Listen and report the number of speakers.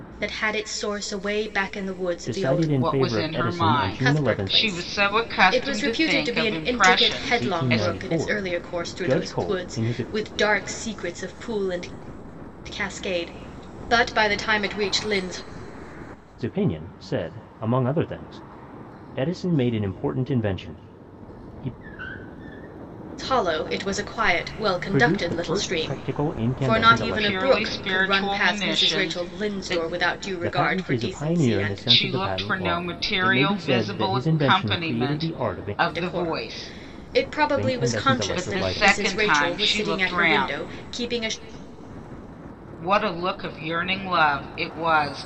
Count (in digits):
3